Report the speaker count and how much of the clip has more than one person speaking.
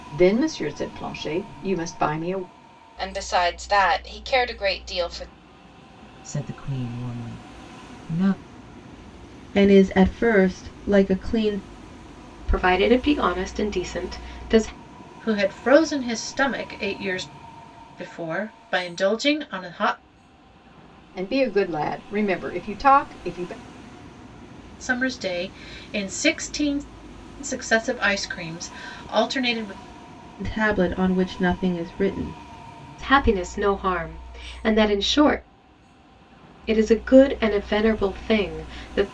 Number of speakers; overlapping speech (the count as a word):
six, no overlap